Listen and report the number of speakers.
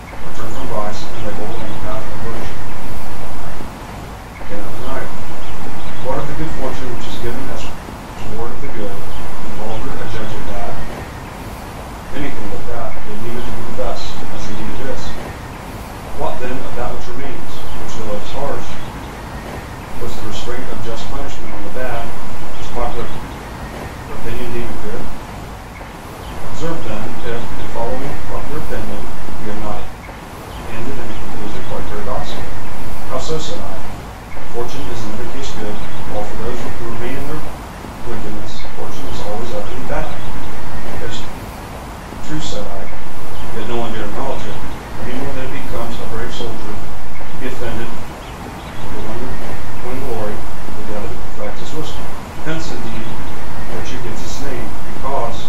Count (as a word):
one